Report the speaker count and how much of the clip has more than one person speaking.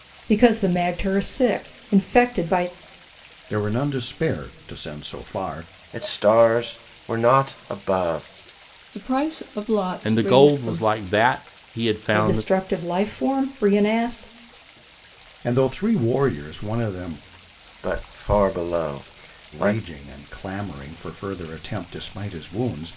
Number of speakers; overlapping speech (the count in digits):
5, about 7%